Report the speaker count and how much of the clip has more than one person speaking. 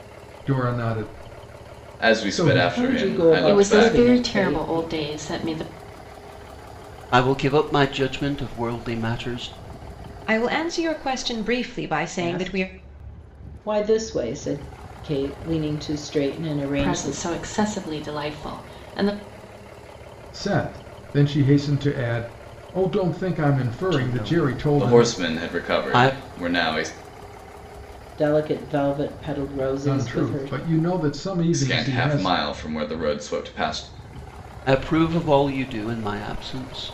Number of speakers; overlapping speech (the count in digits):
6, about 21%